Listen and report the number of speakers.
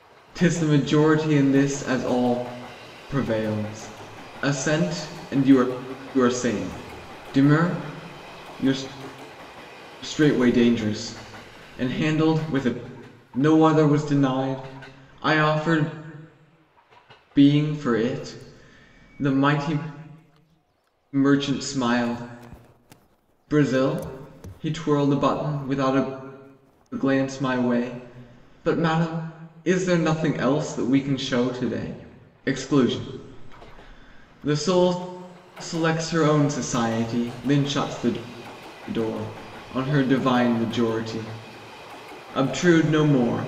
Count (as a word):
one